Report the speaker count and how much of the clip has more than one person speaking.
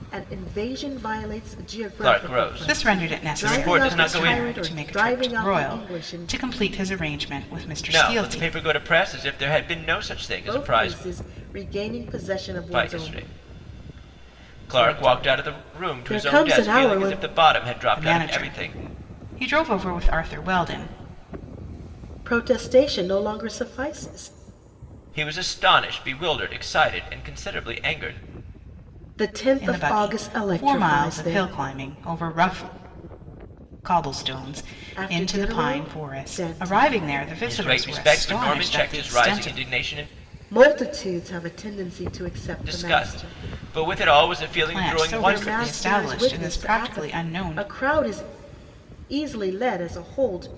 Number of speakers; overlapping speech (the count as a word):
three, about 39%